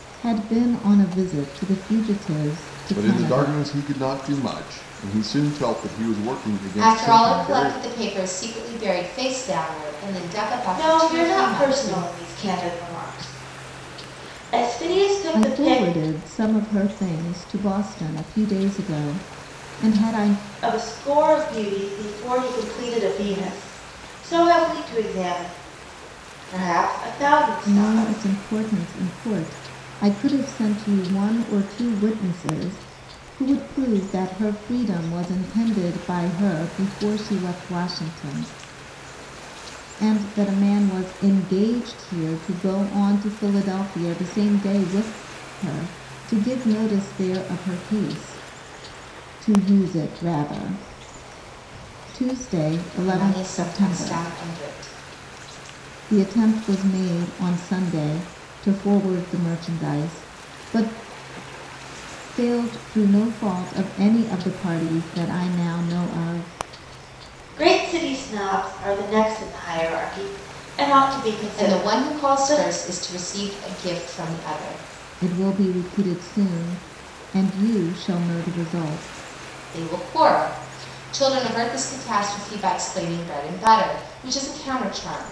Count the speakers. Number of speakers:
4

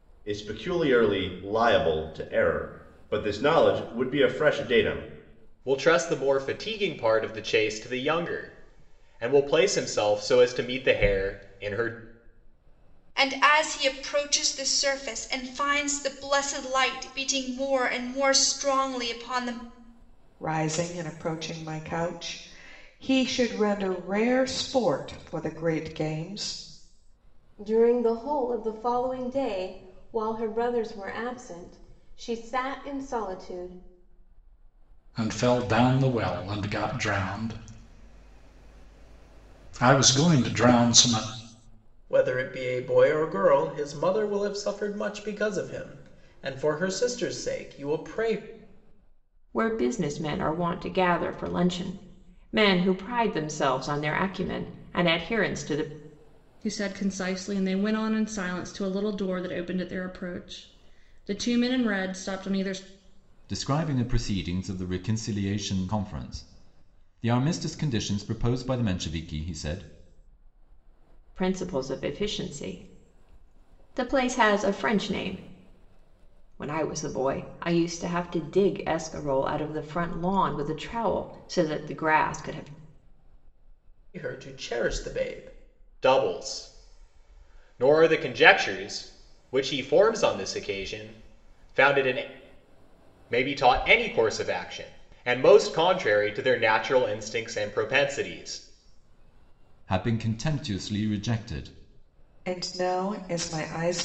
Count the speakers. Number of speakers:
10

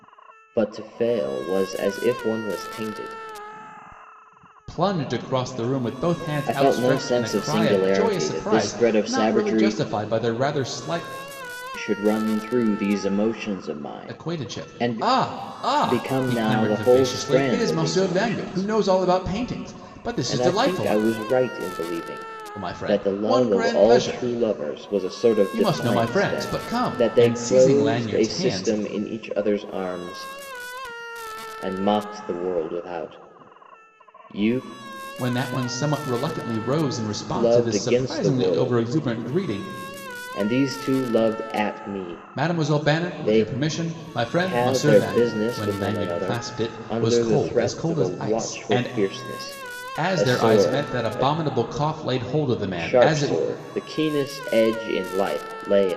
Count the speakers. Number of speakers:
2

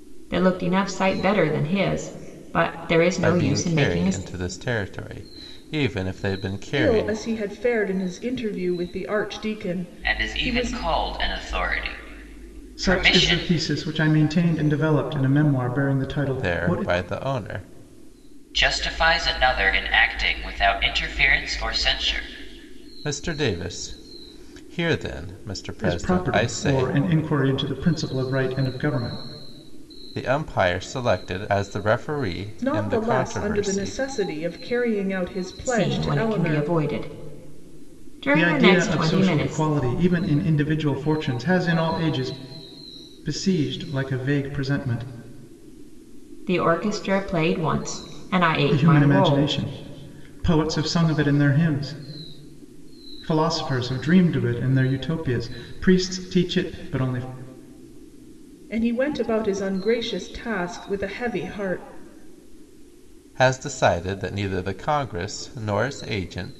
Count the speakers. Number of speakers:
5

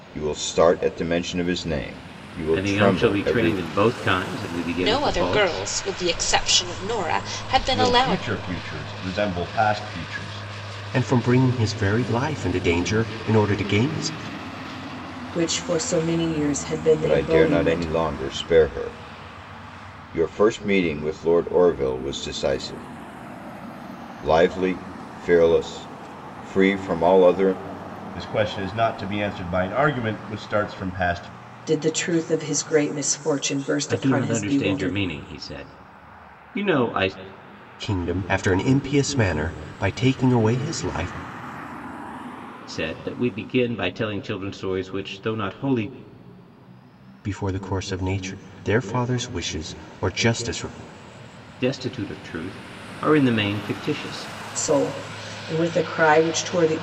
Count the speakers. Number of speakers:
6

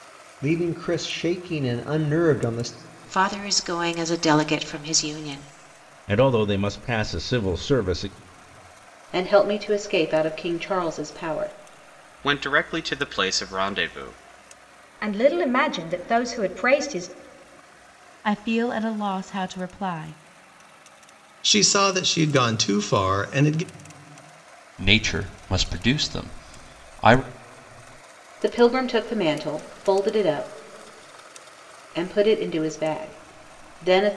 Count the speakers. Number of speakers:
9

